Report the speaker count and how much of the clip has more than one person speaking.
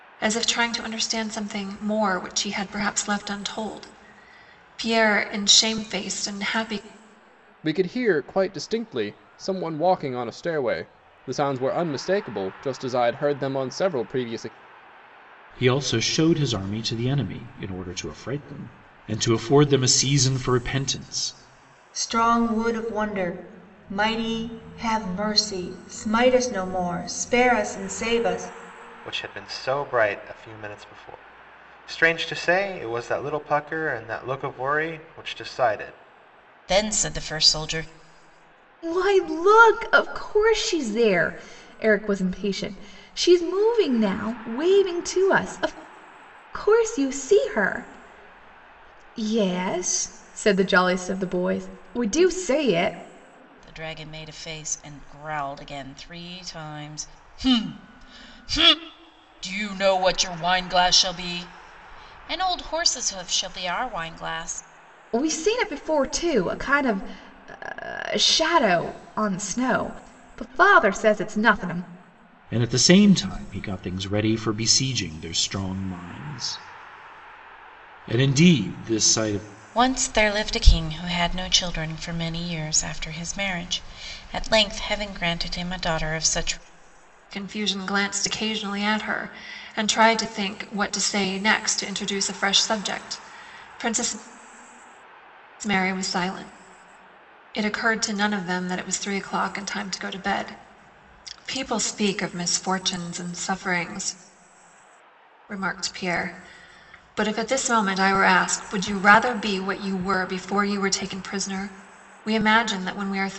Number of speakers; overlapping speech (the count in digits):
7, no overlap